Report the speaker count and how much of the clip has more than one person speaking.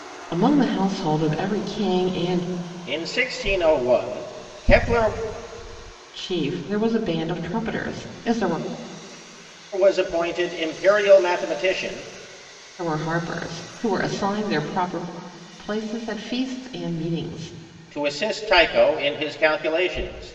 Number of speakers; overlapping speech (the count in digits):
2, no overlap